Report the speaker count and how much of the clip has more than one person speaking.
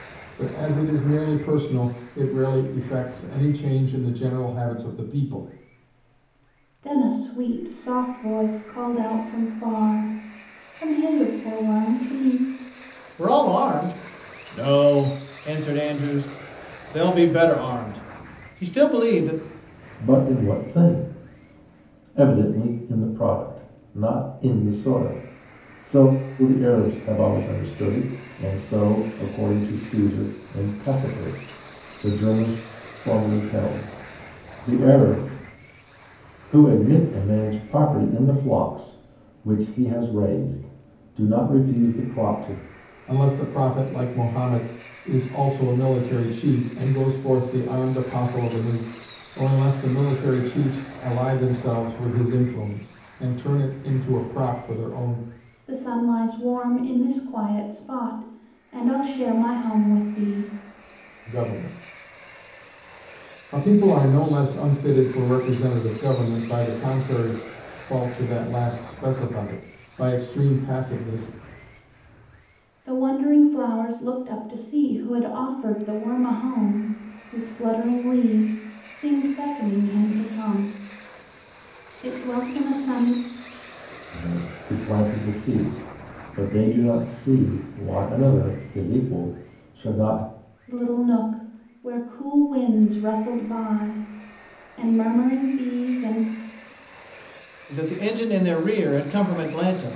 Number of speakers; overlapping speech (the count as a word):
four, no overlap